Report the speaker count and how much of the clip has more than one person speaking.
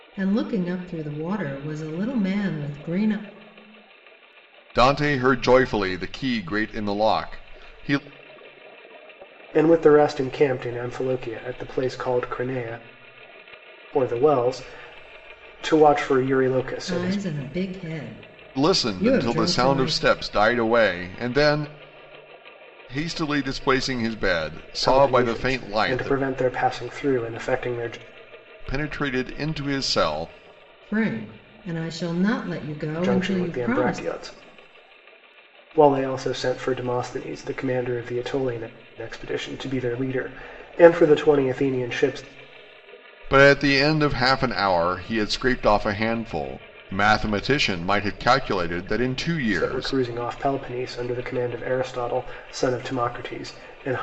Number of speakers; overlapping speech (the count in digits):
3, about 9%